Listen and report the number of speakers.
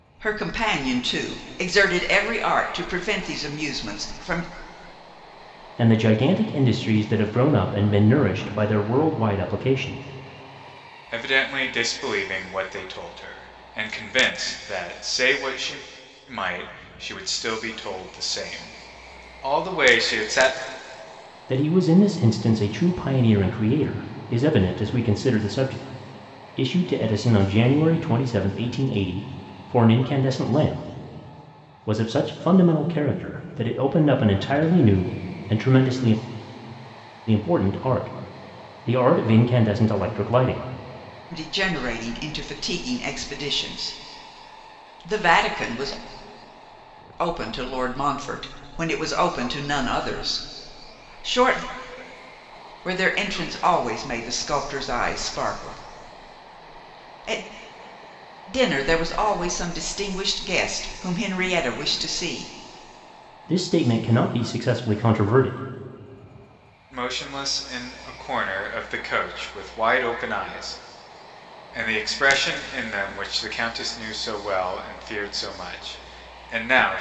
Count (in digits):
3